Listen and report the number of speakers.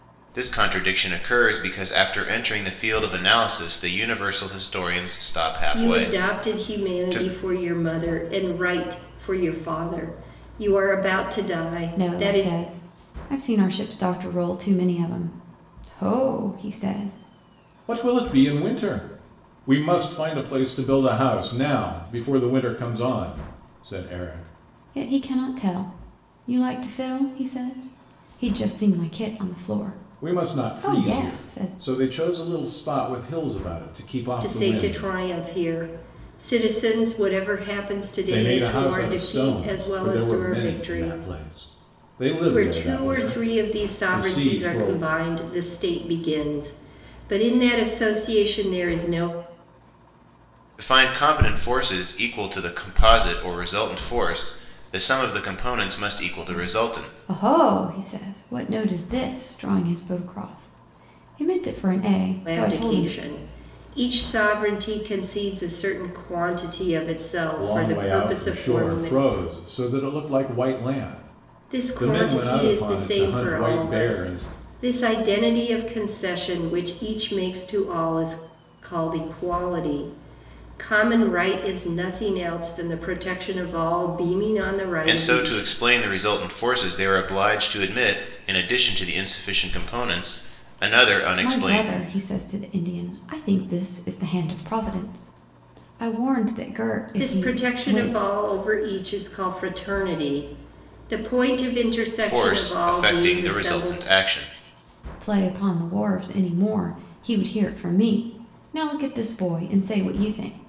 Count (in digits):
4